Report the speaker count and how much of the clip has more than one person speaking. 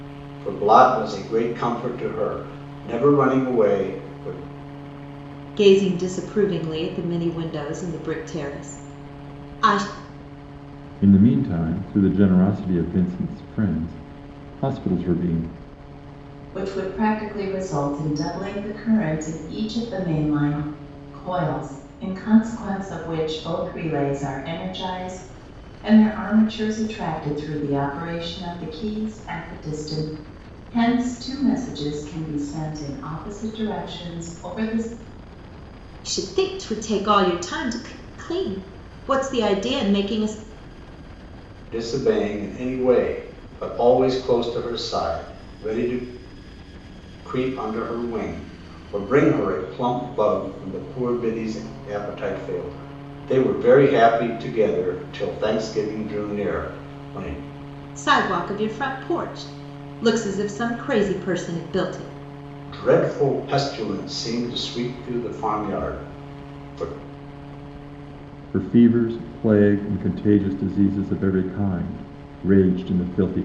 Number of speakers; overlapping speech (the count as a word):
four, no overlap